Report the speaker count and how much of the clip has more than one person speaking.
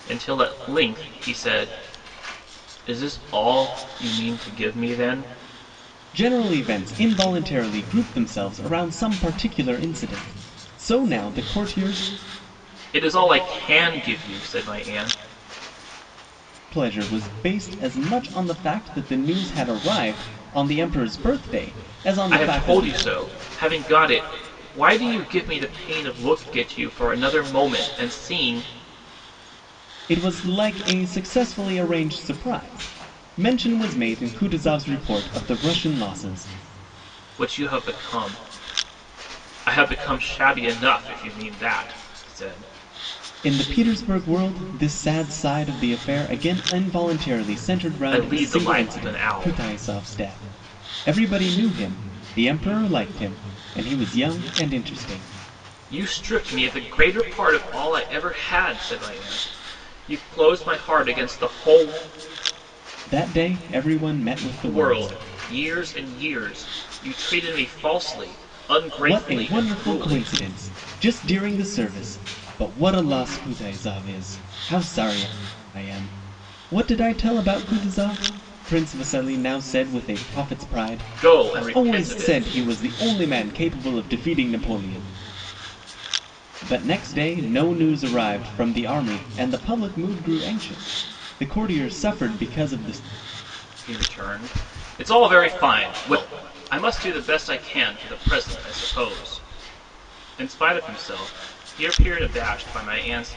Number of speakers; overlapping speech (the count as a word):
two, about 5%